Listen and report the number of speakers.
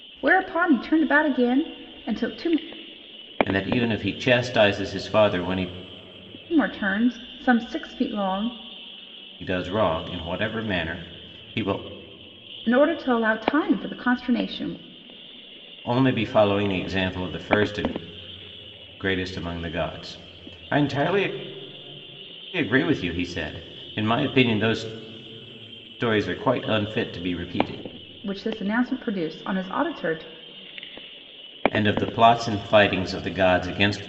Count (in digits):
2